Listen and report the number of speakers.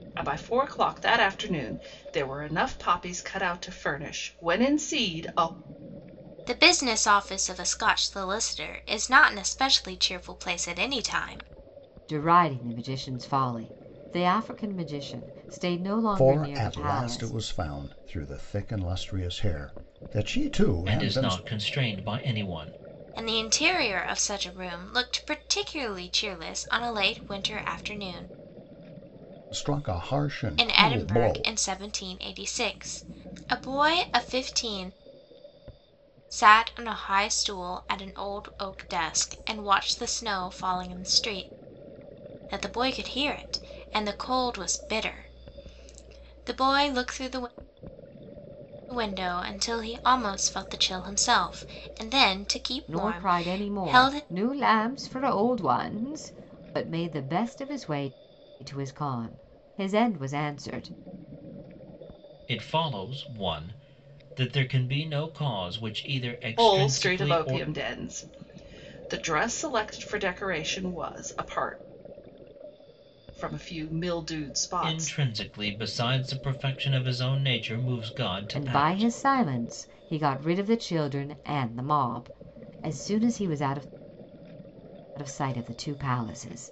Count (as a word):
five